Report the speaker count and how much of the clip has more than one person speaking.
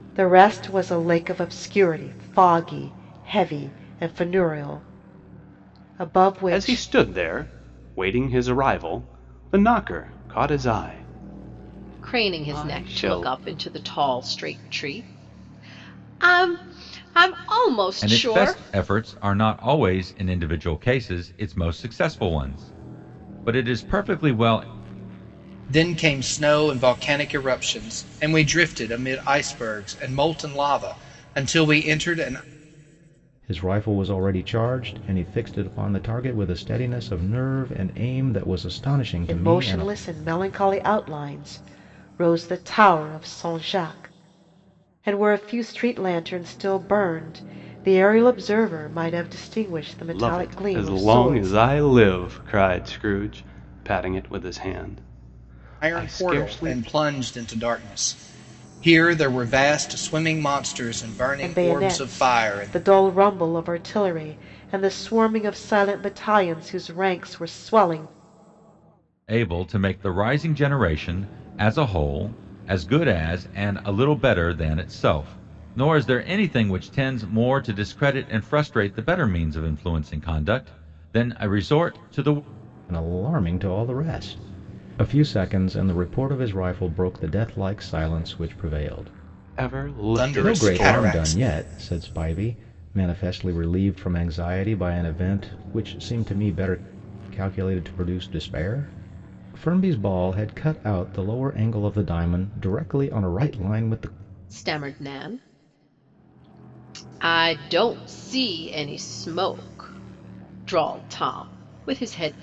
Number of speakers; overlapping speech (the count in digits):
6, about 7%